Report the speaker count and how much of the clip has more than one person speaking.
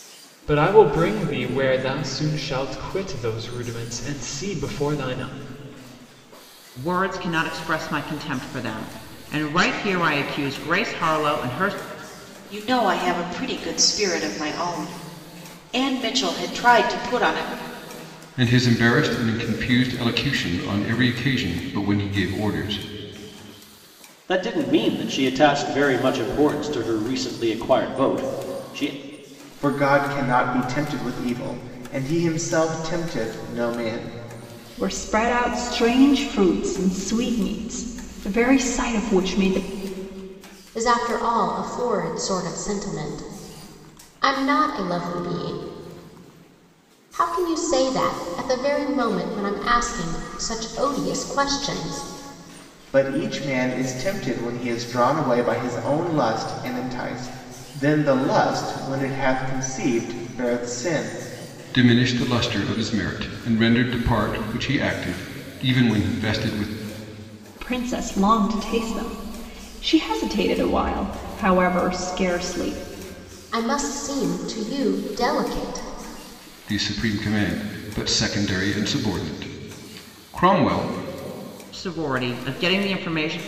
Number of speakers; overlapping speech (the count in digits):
8, no overlap